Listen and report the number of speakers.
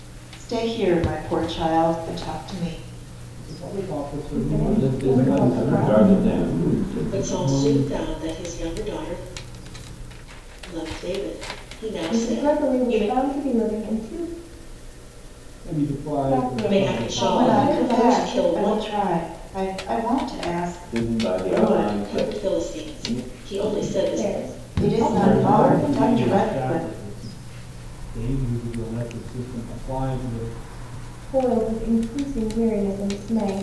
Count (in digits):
7